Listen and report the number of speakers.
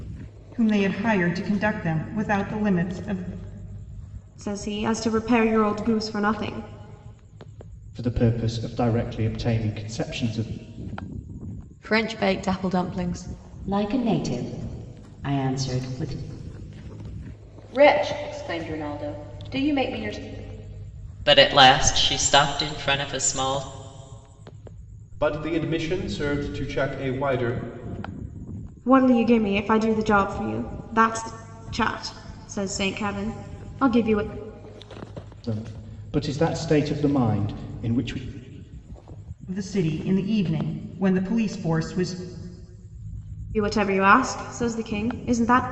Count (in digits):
8